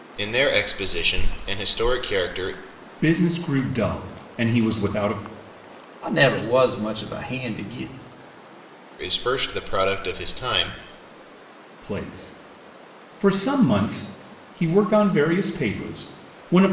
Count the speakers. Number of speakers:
three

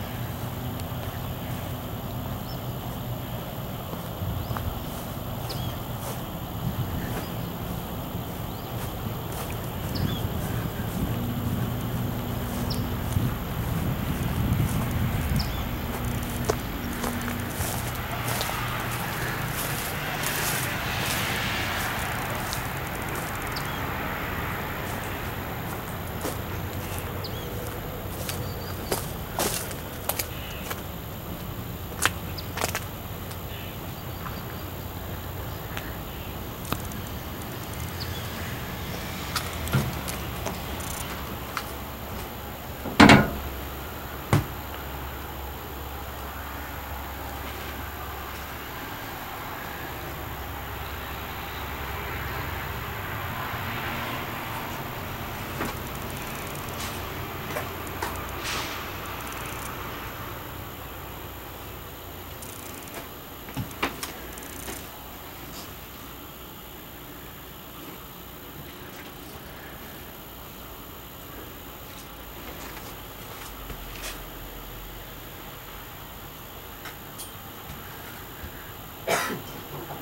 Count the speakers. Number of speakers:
zero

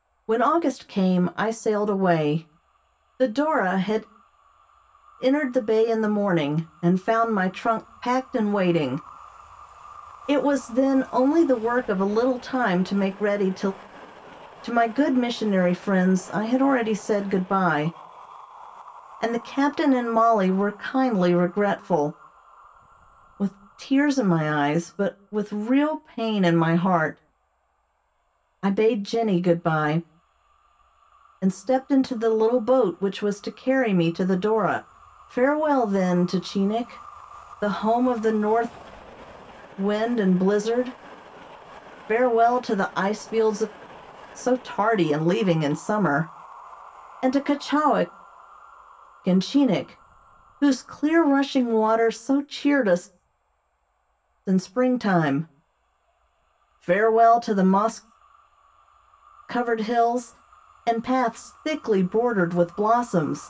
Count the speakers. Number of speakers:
one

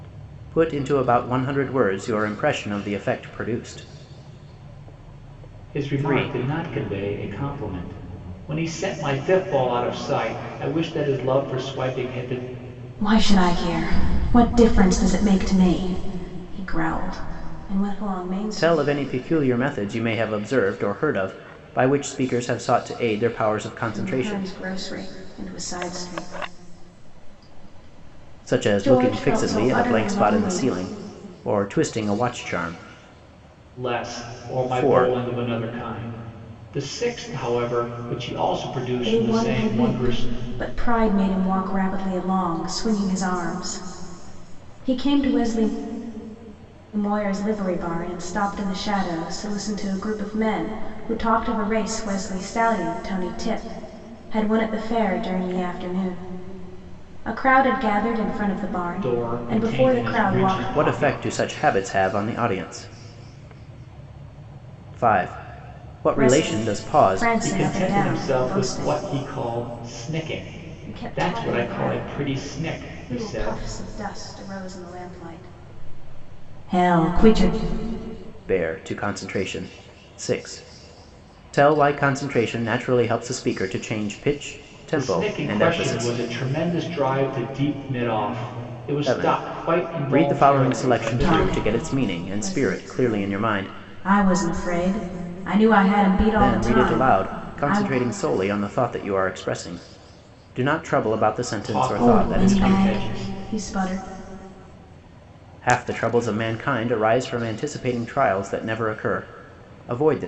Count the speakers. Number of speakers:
three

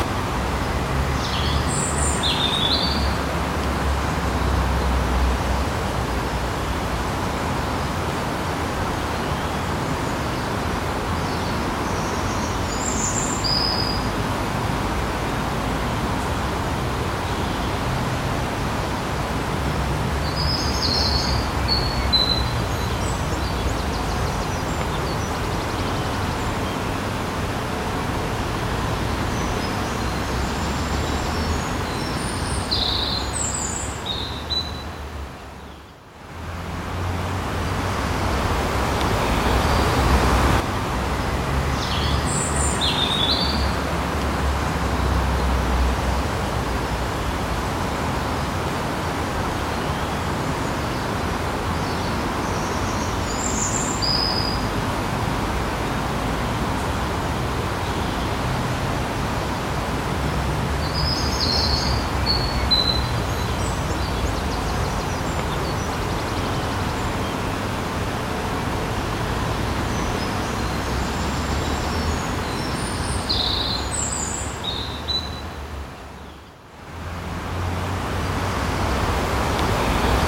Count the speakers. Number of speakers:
zero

